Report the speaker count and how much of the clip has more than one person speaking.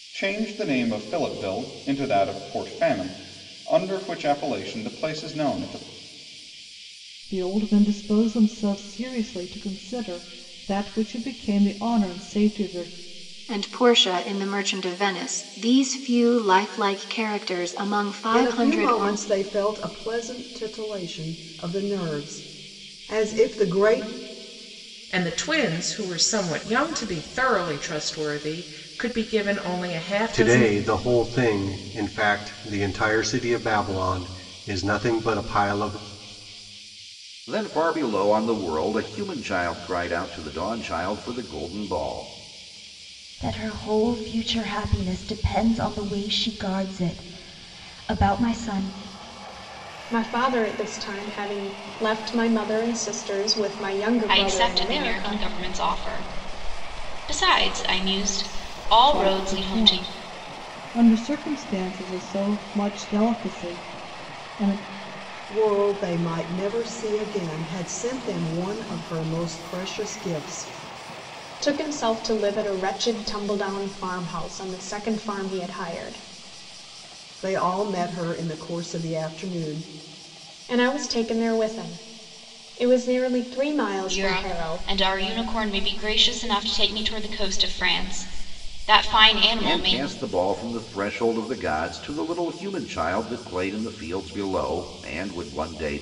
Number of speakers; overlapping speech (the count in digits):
10, about 5%